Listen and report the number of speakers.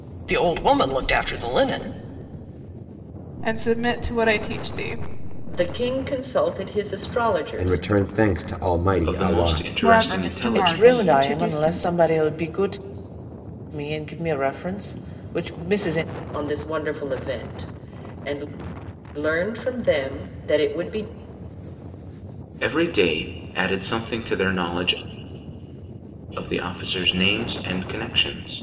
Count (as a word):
seven